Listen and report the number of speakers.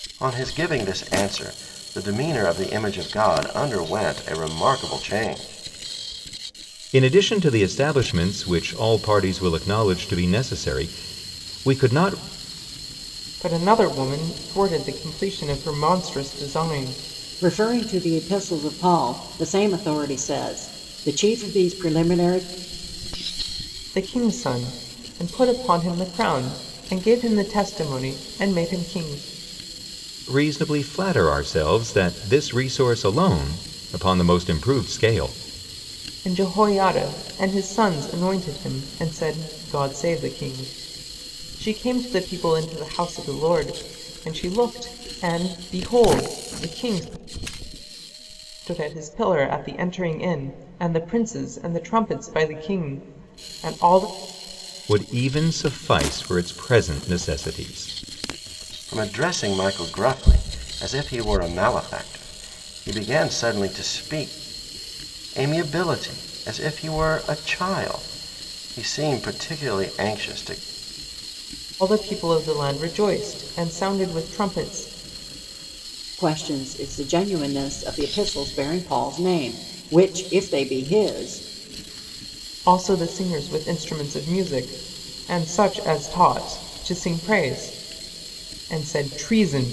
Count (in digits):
4